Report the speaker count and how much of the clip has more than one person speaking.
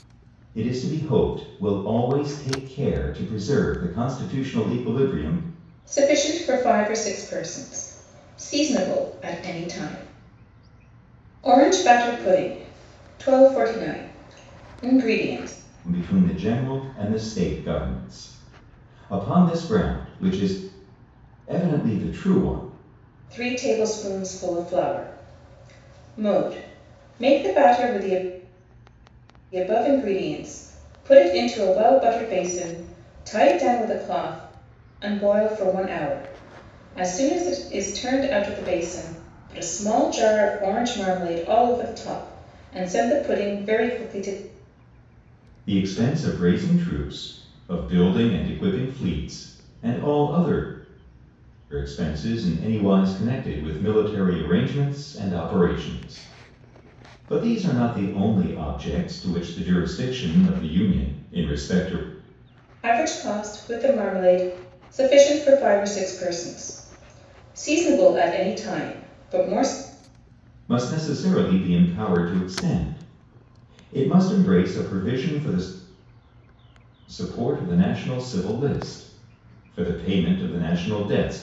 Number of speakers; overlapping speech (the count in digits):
2, no overlap